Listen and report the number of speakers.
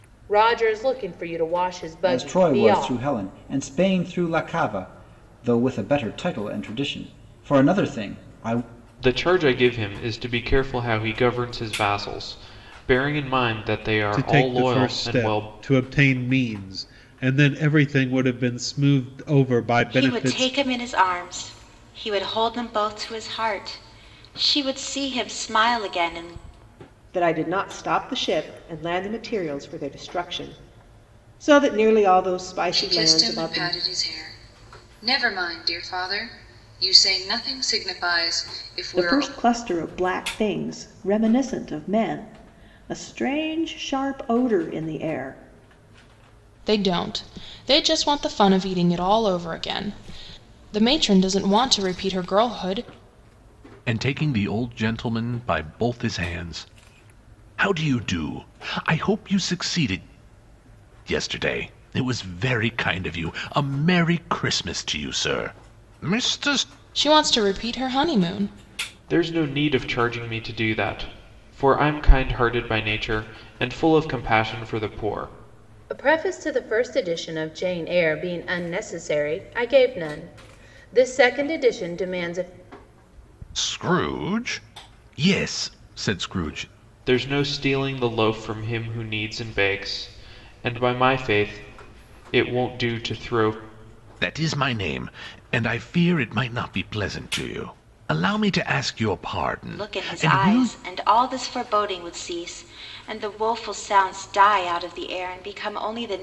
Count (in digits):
10